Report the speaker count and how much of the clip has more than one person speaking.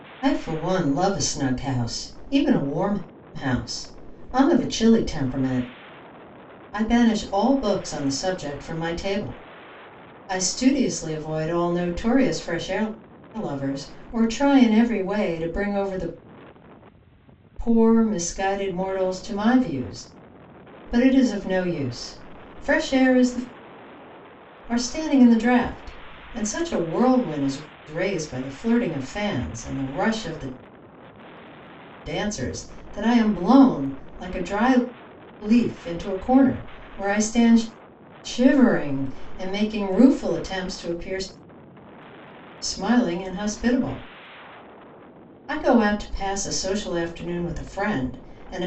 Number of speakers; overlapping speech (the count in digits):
1, no overlap